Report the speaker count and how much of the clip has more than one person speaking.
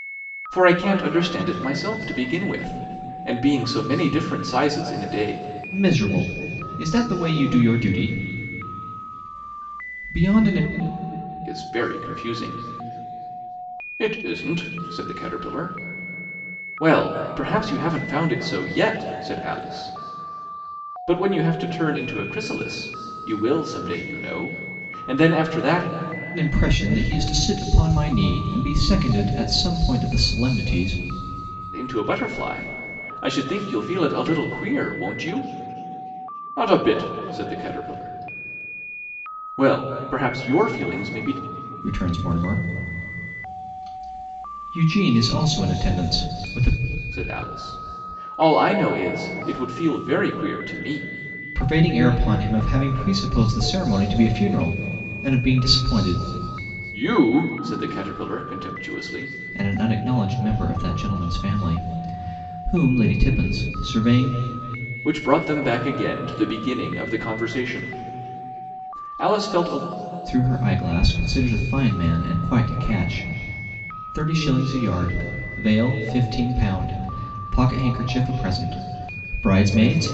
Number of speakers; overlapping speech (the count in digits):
2, no overlap